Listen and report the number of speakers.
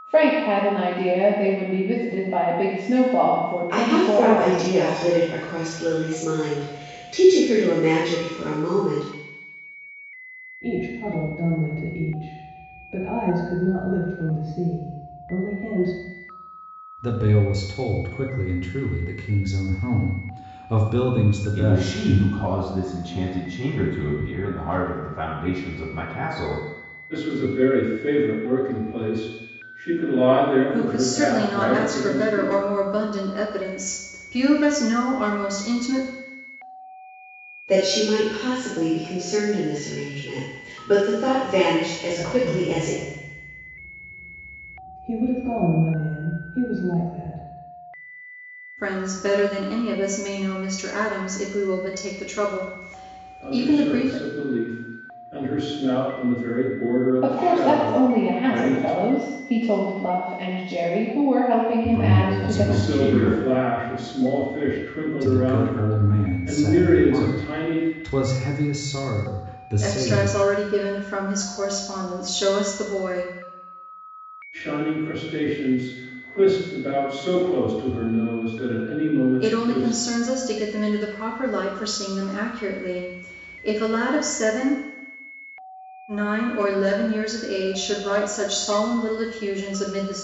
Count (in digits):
7